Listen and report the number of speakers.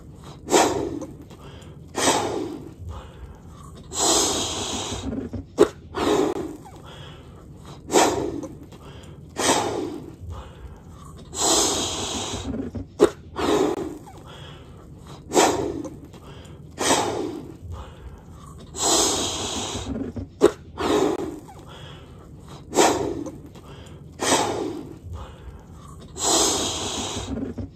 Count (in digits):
0